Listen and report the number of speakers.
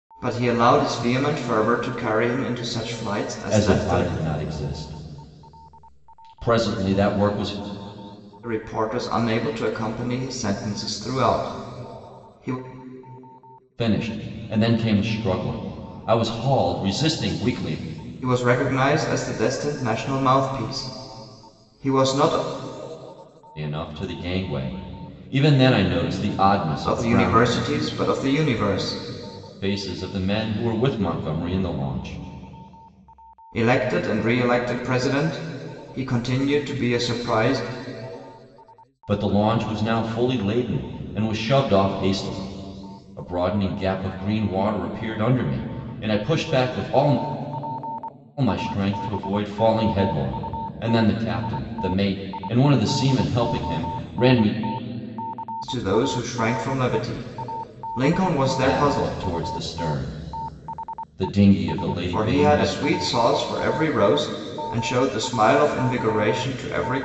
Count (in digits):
2